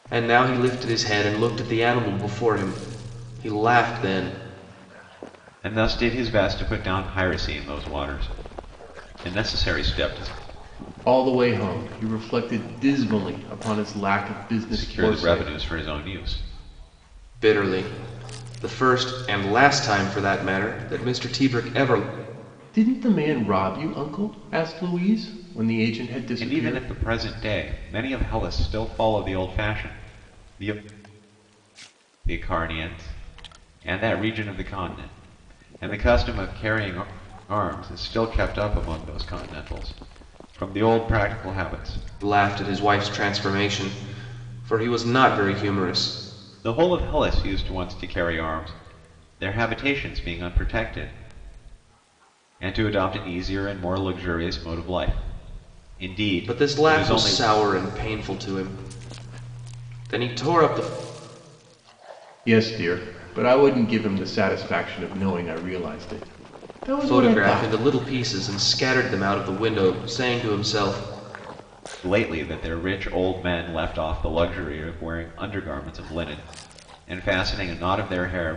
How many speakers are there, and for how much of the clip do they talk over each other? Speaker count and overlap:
3, about 4%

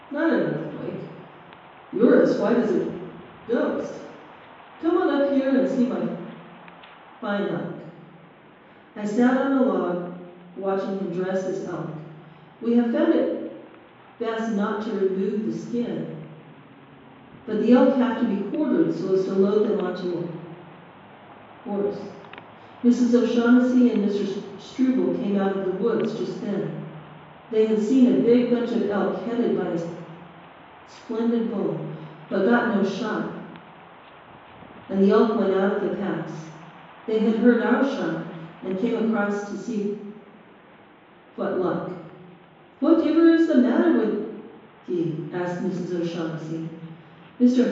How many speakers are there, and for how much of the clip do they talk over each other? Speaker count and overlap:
1, no overlap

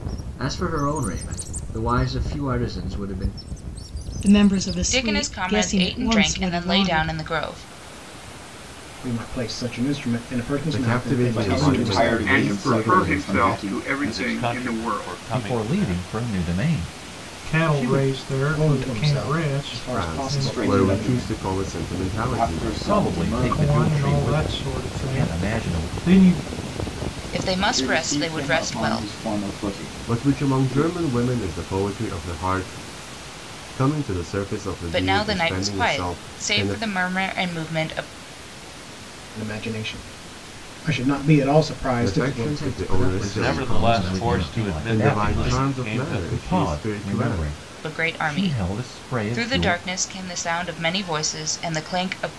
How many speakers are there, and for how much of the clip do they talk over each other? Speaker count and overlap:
10, about 53%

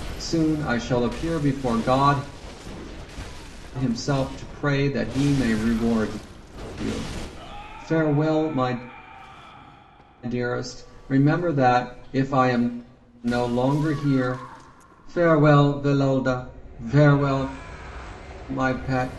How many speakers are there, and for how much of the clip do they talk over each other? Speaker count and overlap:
1, no overlap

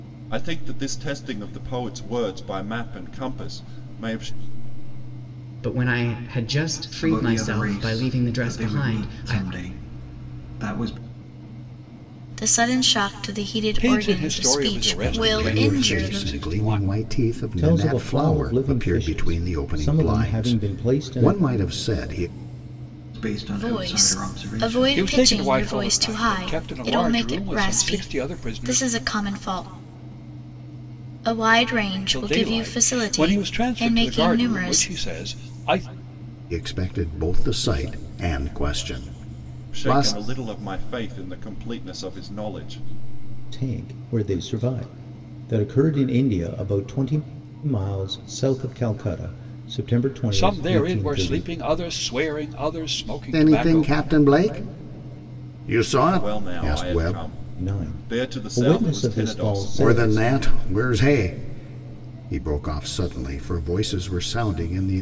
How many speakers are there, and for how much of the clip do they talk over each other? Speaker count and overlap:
7, about 37%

